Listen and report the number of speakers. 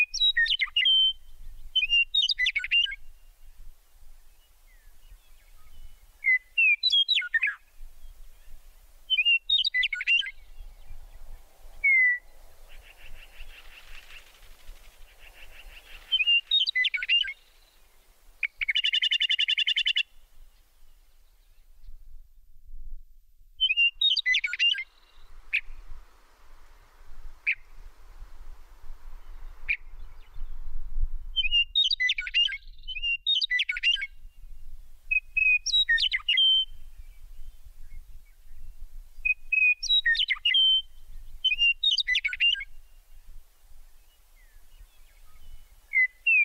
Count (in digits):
0